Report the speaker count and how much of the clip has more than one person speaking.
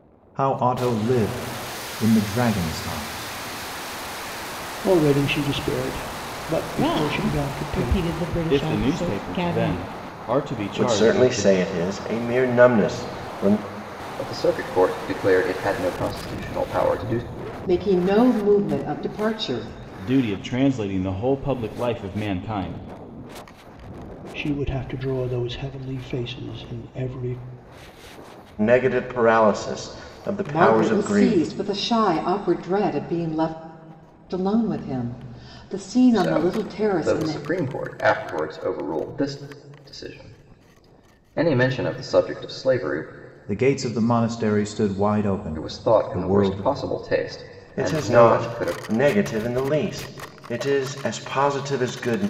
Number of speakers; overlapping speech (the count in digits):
7, about 15%